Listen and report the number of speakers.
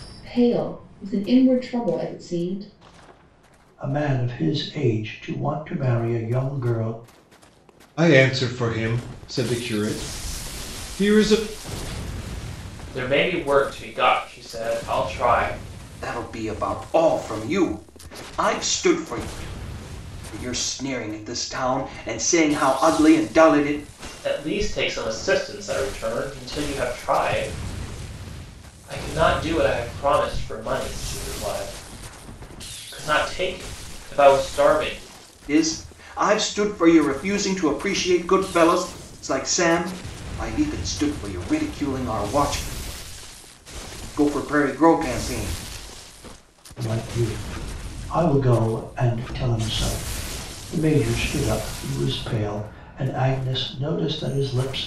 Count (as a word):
five